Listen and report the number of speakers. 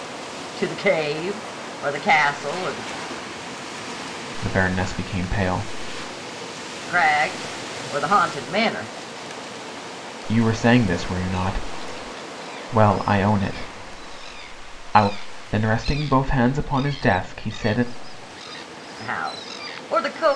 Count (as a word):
two